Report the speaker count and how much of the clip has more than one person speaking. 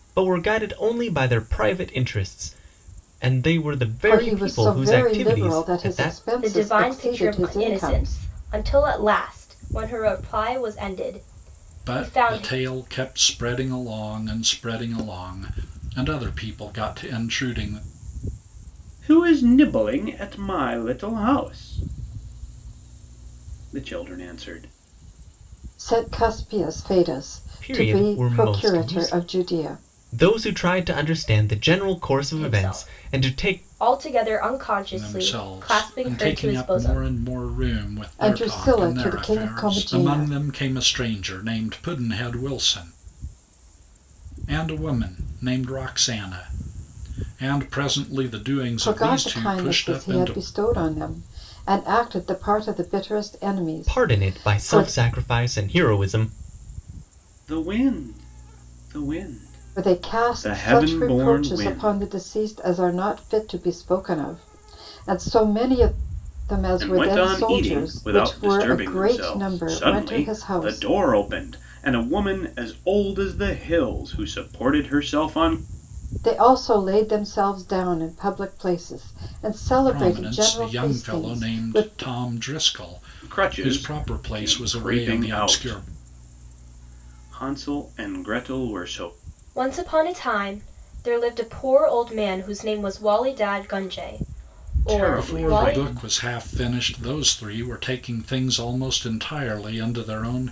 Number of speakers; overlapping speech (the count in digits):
5, about 28%